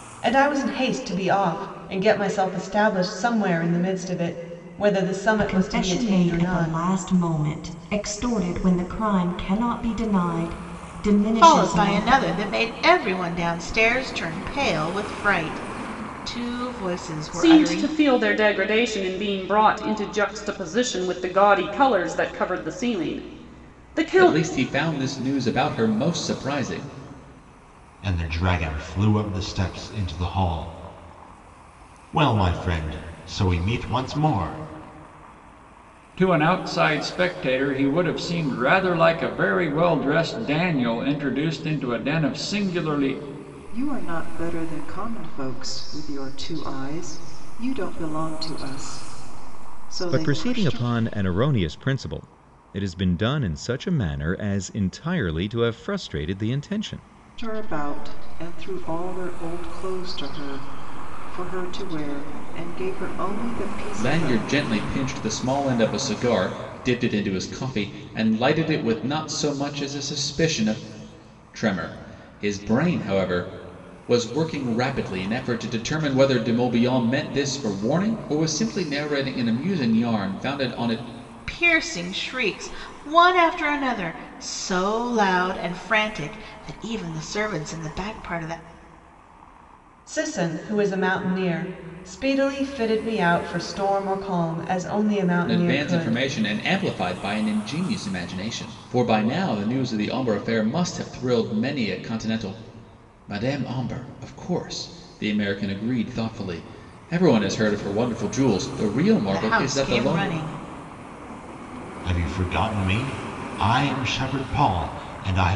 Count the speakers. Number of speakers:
9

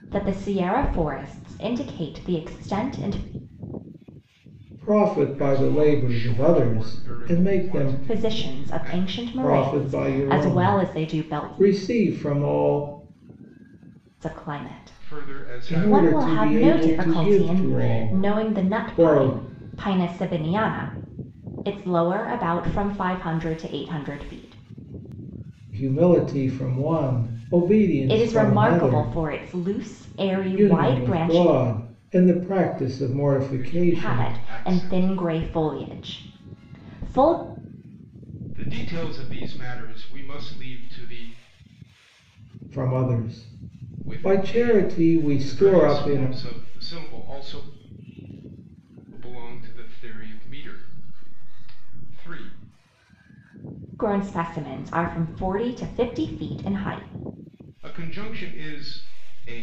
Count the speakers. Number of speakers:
3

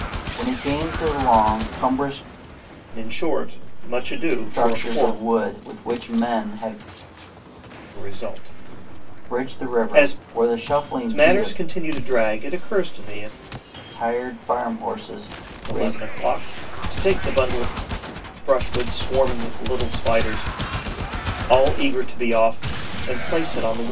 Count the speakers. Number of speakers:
2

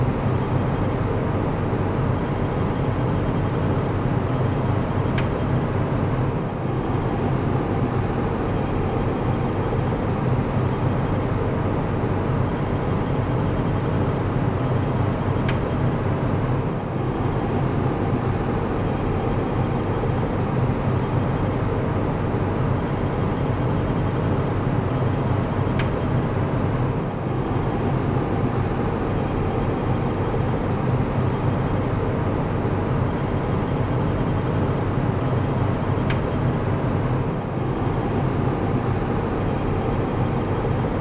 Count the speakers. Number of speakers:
0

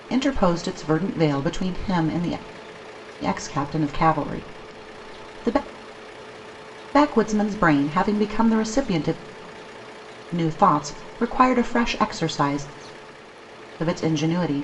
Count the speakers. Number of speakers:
1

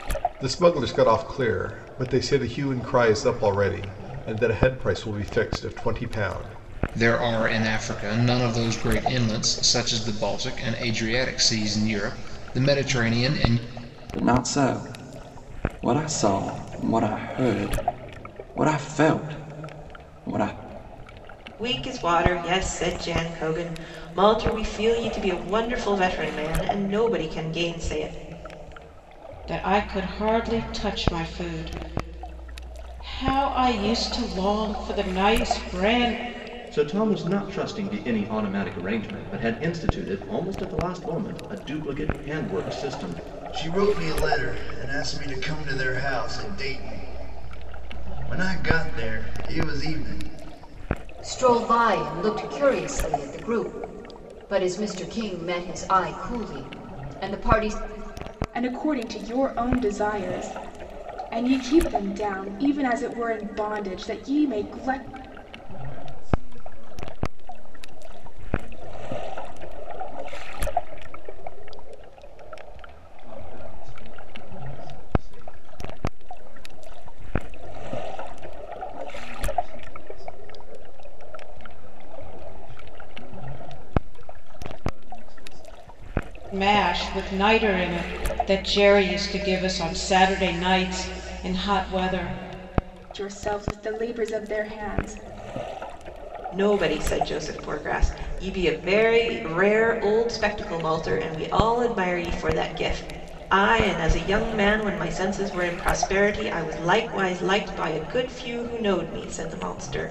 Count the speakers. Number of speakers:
10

